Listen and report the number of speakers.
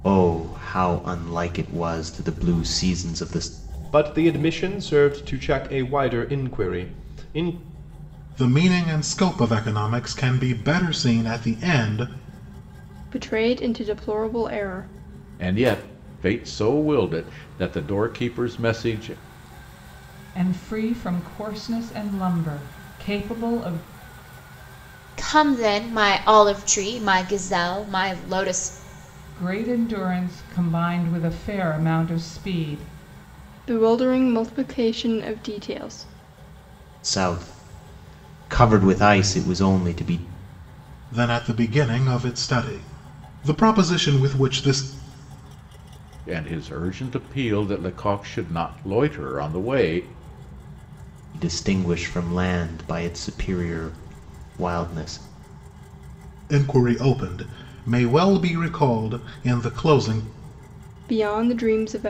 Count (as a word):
seven